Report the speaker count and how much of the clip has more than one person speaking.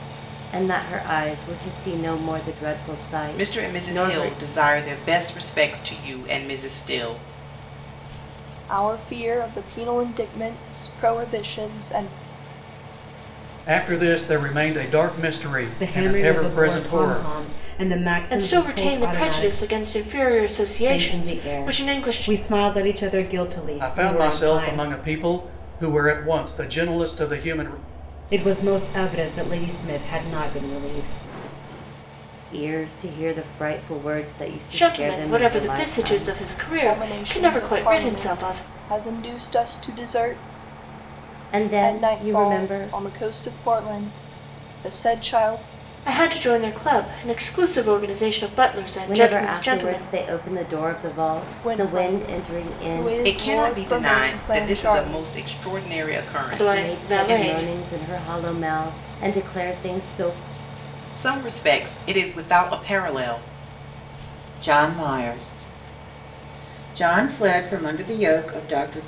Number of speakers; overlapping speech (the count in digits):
6, about 25%